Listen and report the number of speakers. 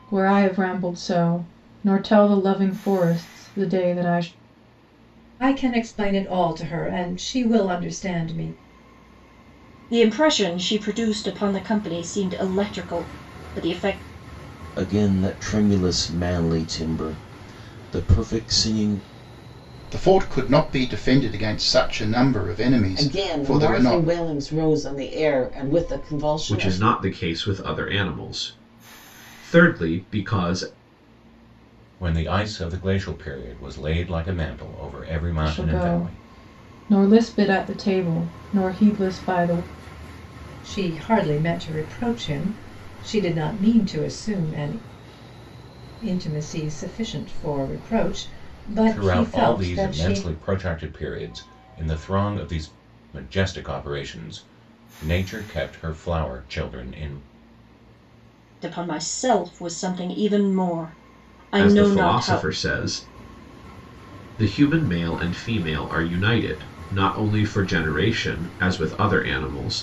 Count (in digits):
8